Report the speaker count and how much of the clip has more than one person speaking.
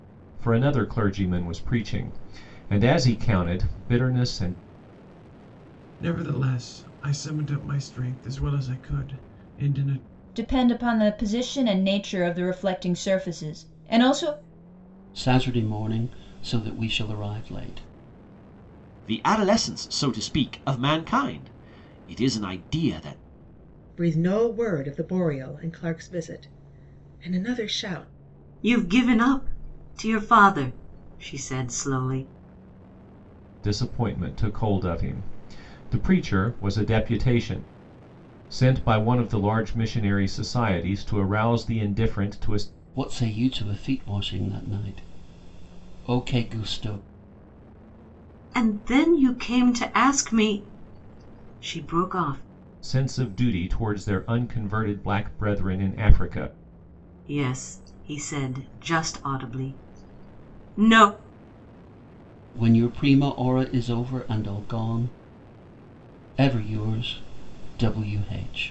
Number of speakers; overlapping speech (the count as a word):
seven, no overlap